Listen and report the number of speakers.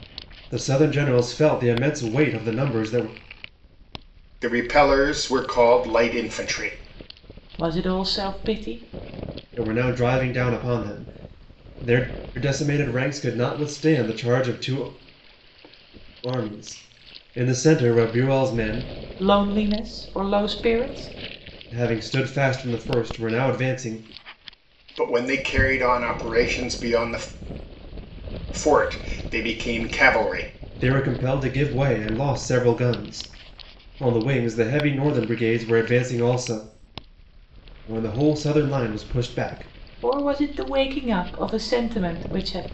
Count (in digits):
3